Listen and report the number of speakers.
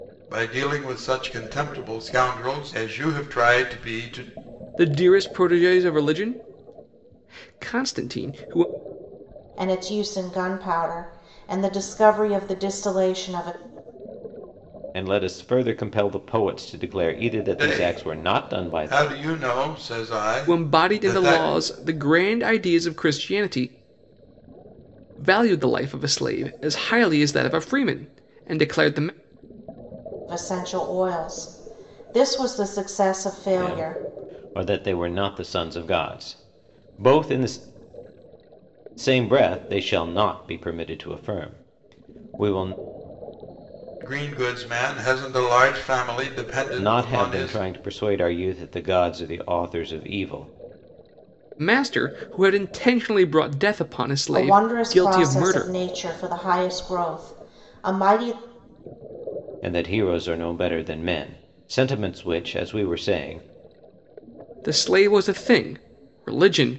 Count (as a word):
four